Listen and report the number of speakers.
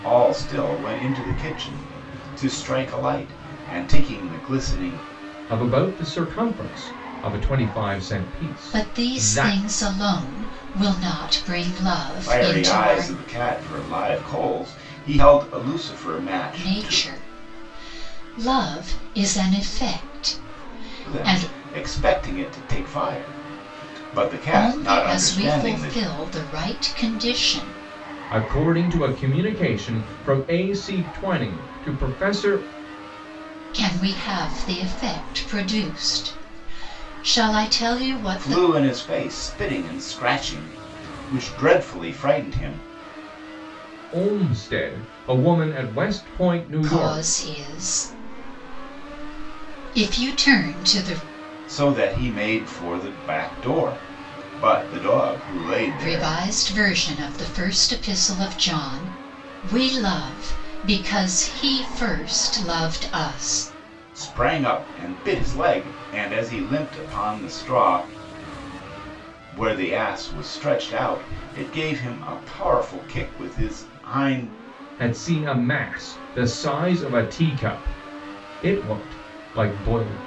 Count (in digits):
3